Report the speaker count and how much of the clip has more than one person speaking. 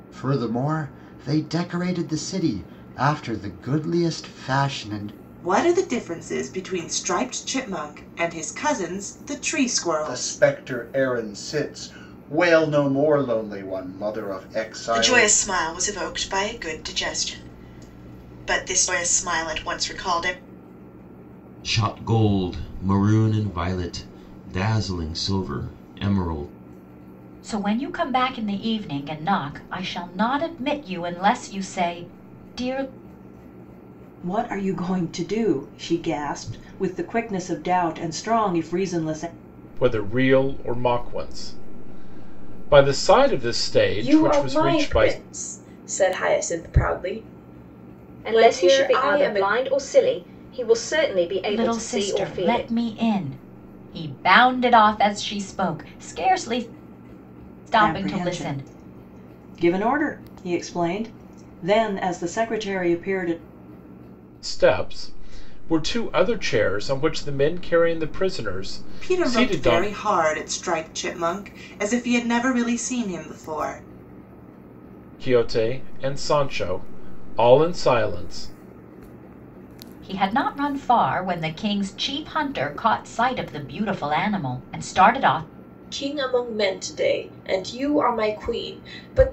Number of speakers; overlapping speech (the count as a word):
ten, about 7%